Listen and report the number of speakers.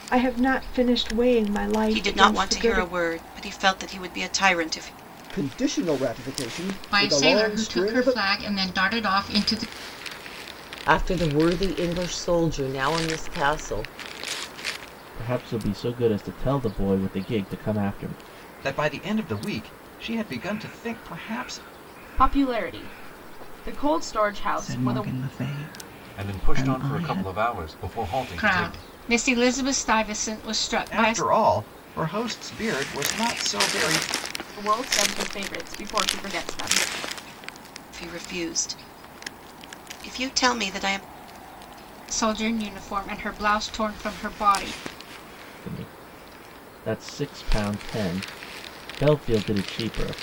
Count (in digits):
10